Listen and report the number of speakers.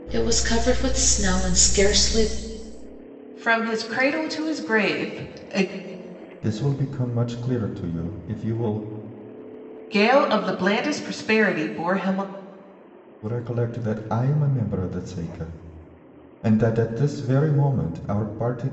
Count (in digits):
3